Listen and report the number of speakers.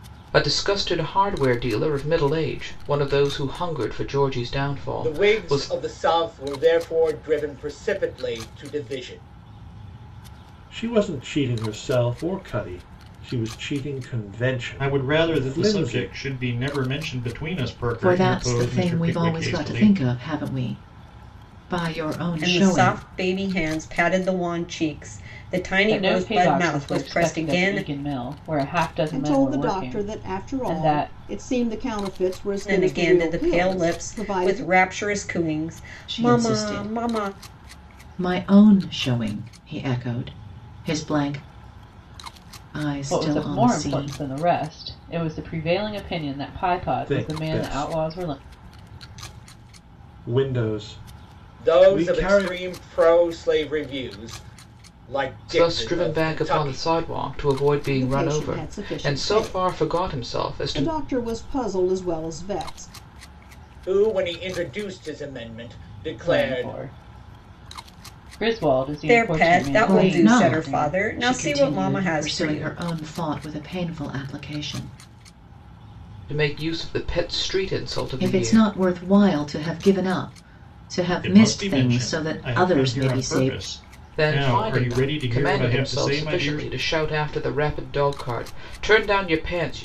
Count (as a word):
eight